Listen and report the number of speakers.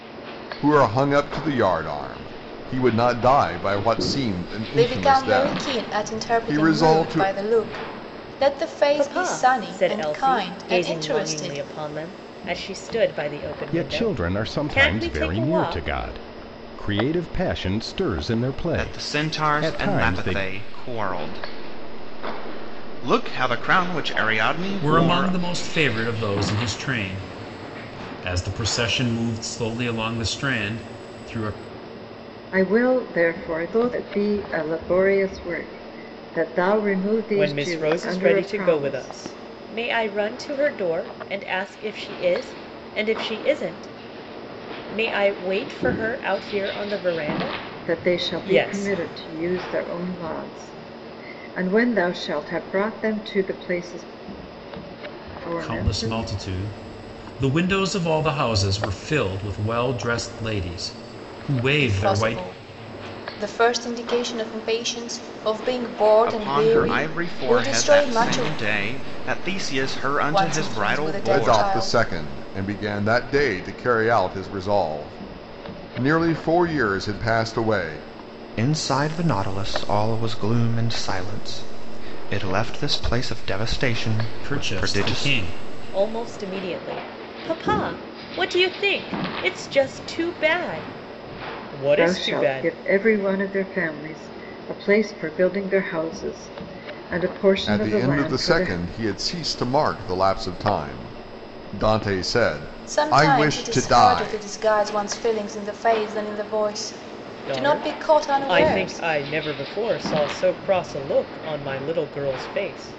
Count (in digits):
7